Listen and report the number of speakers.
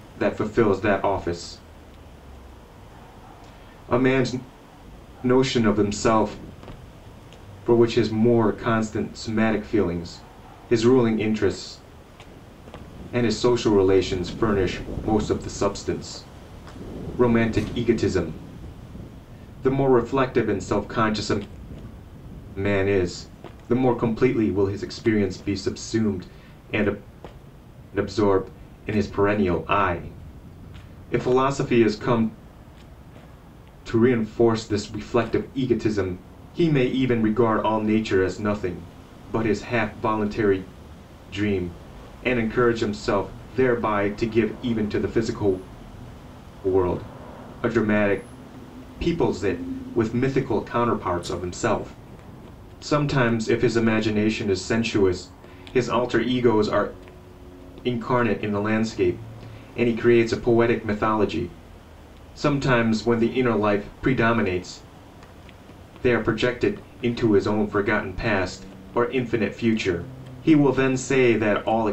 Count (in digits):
1